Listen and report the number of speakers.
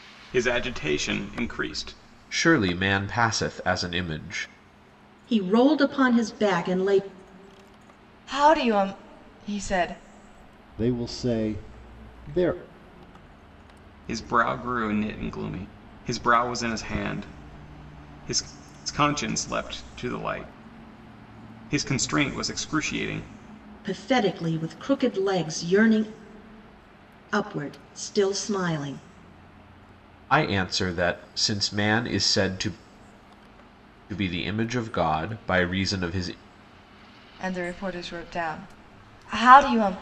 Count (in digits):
5